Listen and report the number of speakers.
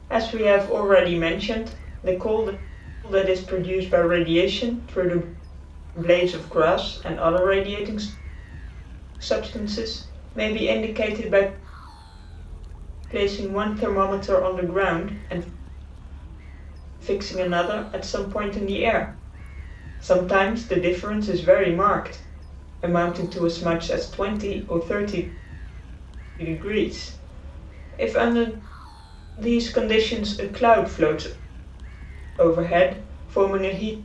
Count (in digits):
1